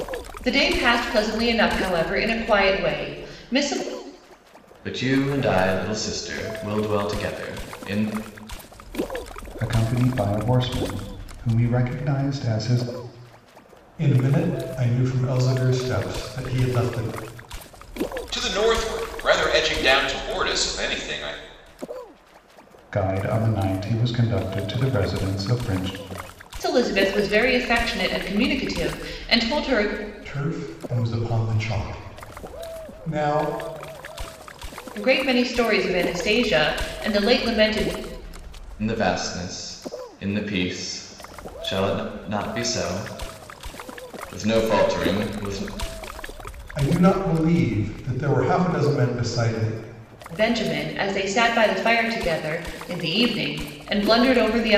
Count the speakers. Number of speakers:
5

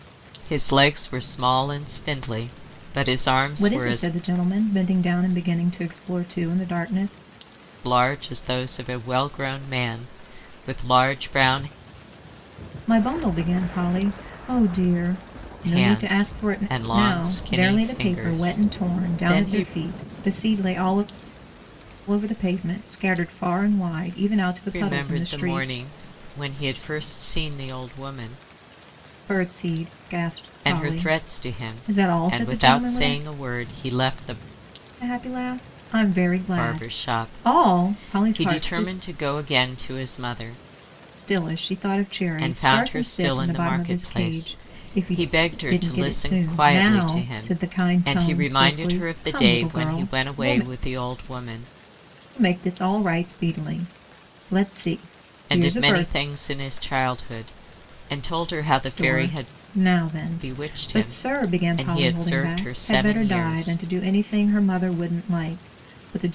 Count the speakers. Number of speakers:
2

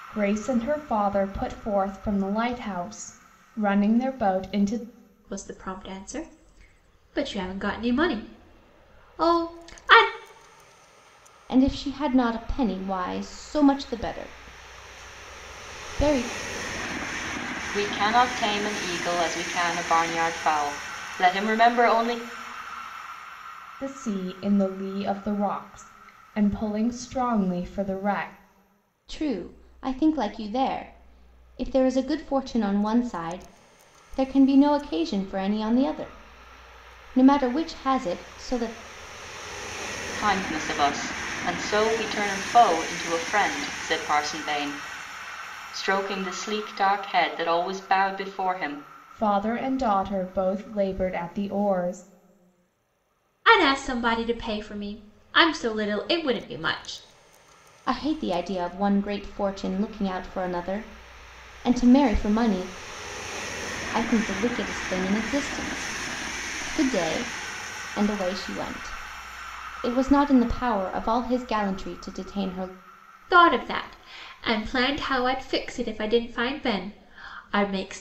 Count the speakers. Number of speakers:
4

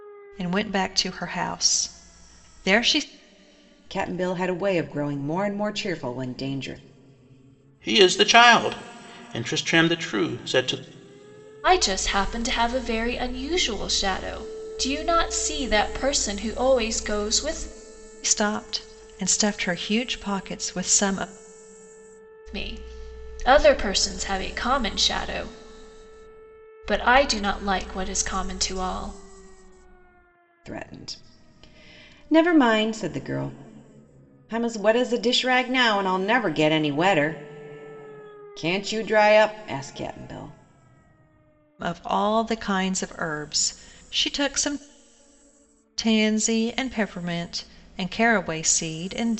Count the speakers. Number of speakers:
4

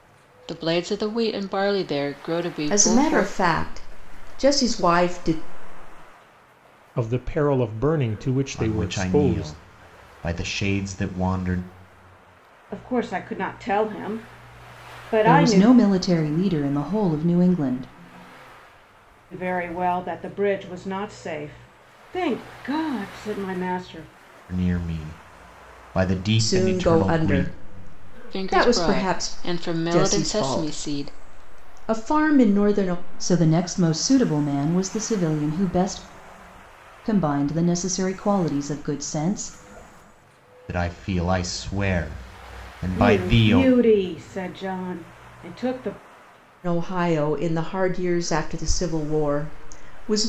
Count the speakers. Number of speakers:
6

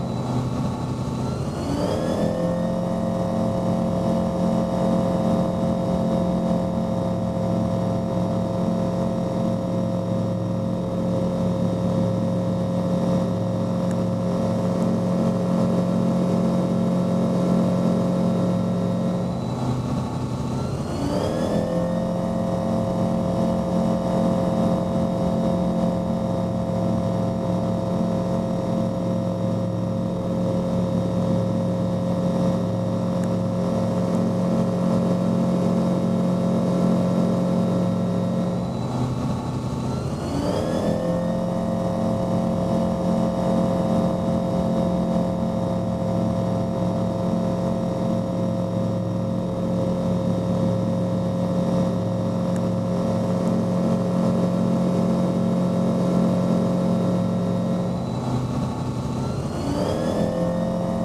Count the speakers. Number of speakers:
0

